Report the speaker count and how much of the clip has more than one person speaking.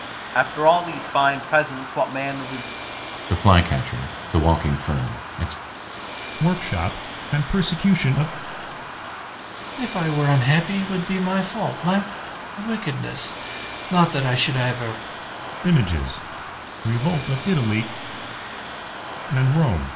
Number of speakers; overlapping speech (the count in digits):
4, no overlap